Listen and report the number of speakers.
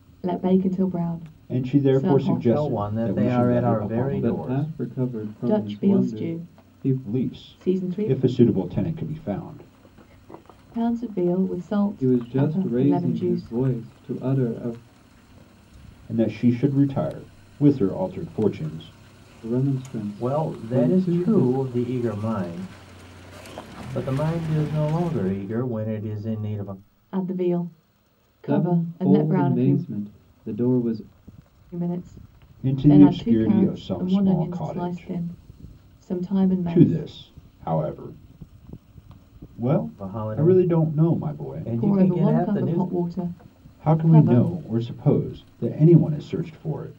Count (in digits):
4